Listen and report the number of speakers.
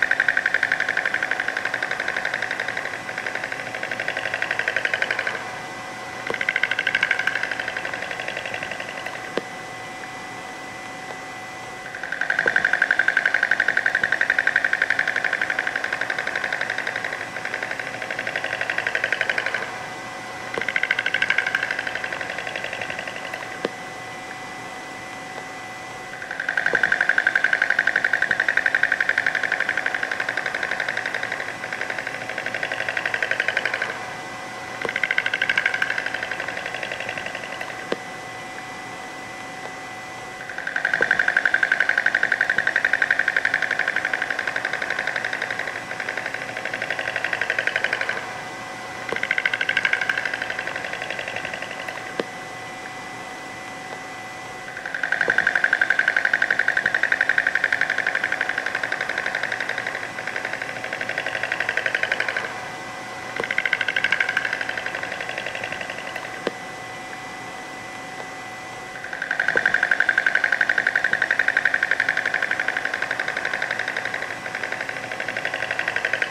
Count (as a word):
zero